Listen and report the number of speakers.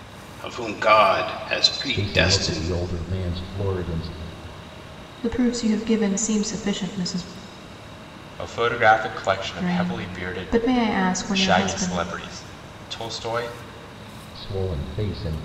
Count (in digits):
4